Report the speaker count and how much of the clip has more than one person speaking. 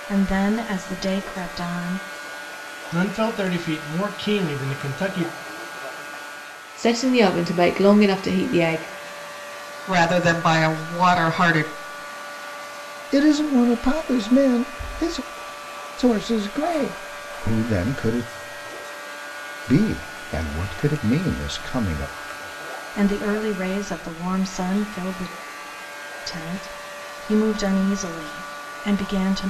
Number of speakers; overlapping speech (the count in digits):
5, no overlap